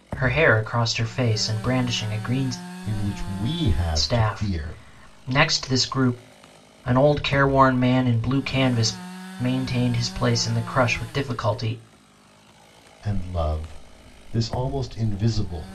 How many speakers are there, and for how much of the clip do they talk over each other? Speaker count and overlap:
two, about 5%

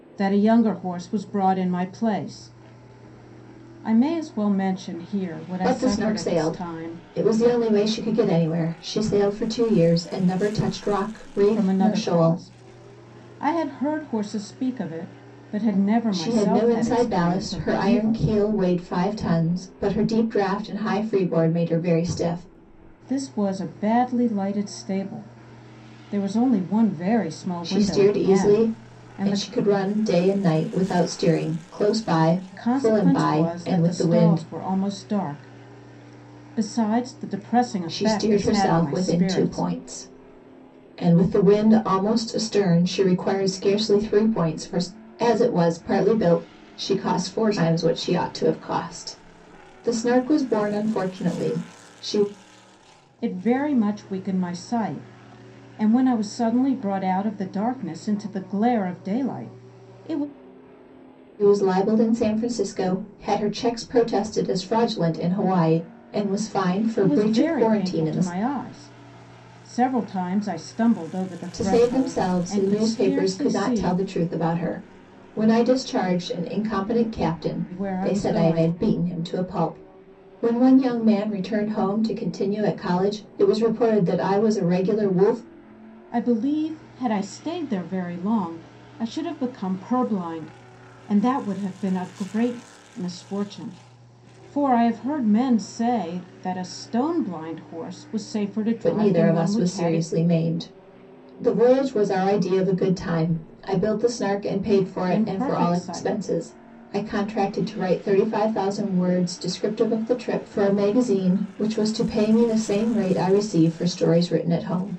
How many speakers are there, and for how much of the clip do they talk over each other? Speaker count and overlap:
two, about 15%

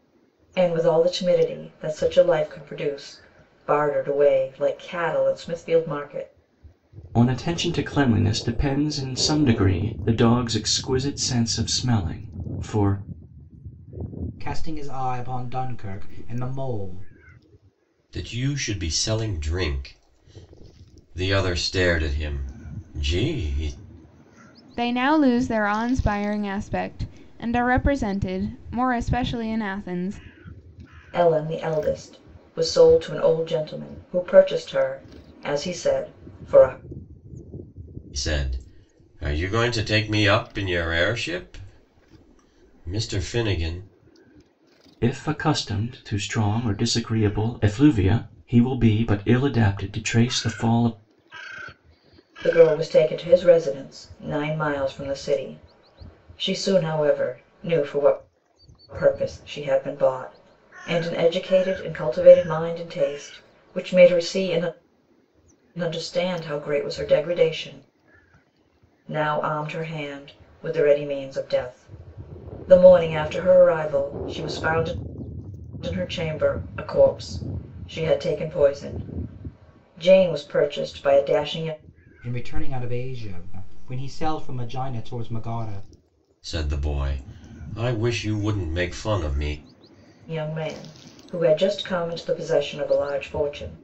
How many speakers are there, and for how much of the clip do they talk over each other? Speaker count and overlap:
five, no overlap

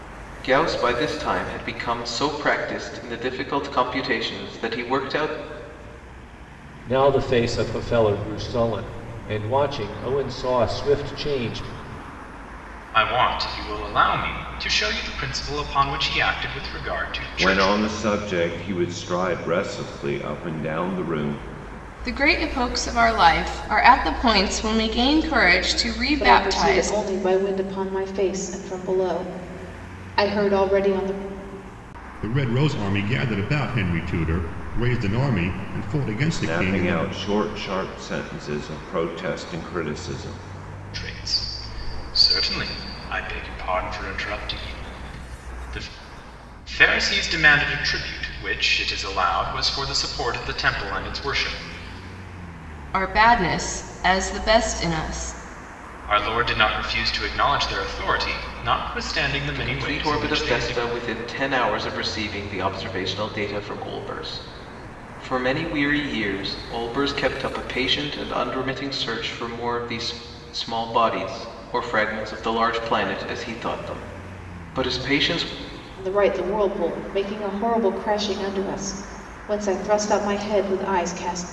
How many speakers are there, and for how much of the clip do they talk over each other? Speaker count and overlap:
seven, about 4%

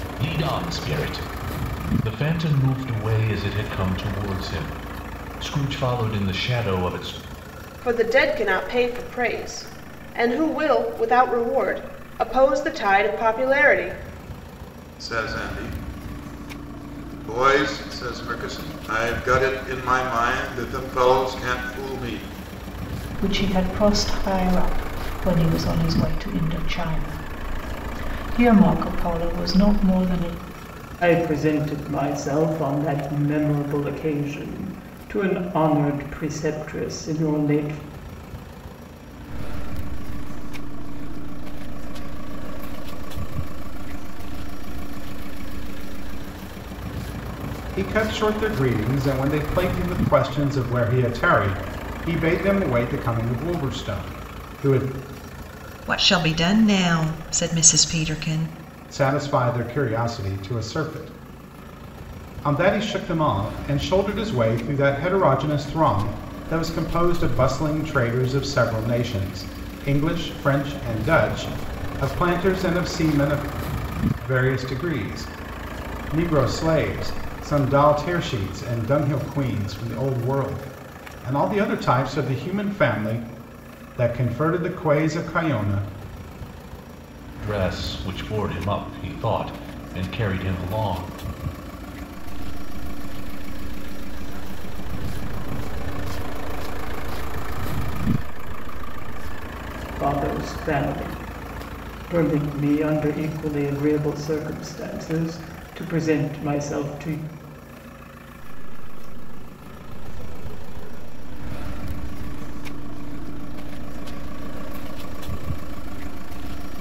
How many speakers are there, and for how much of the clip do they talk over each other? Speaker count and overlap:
eight, no overlap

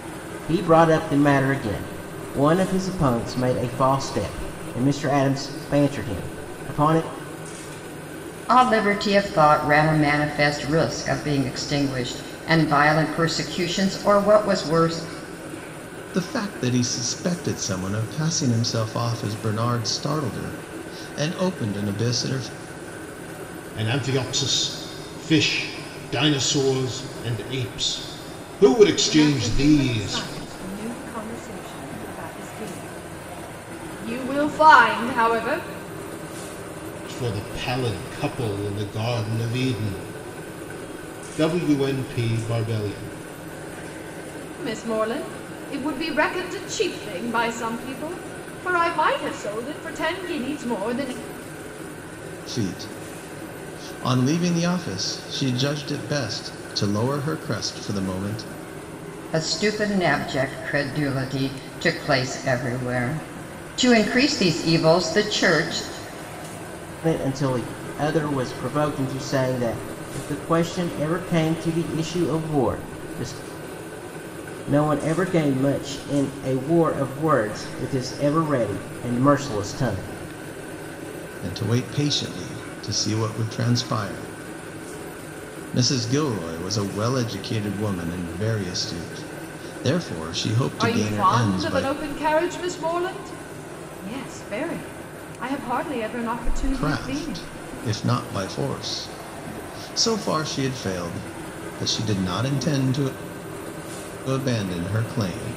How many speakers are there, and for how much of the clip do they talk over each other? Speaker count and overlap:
five, about 3%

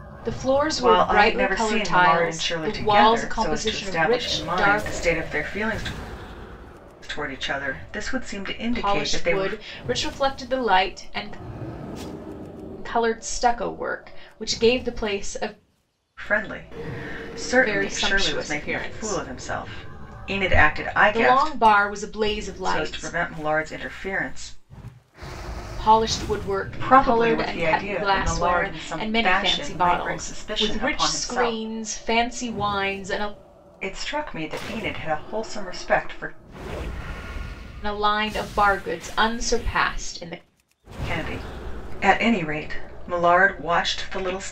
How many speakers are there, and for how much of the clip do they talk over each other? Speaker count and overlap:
two, about 28%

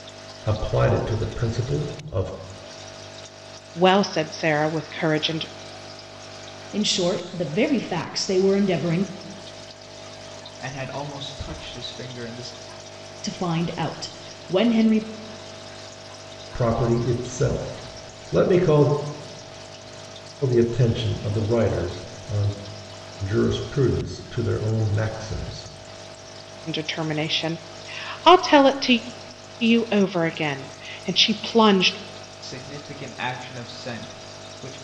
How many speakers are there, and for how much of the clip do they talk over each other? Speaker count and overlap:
four, no overlap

